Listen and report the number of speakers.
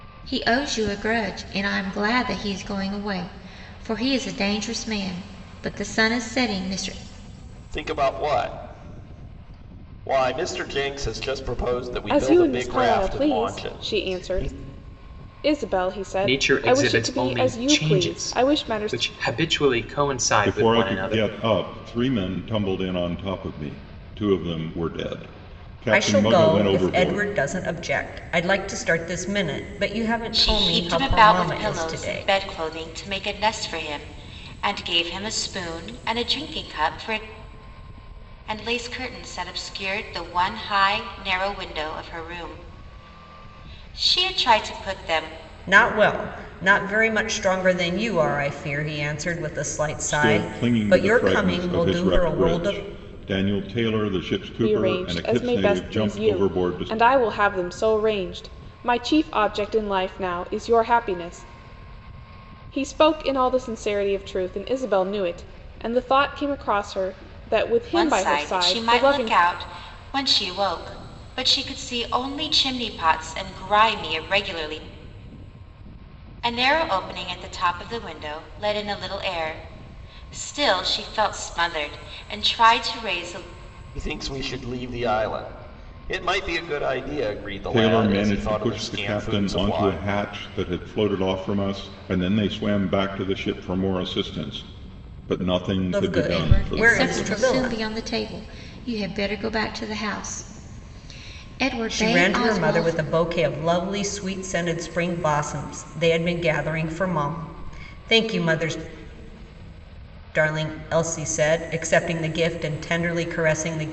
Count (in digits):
7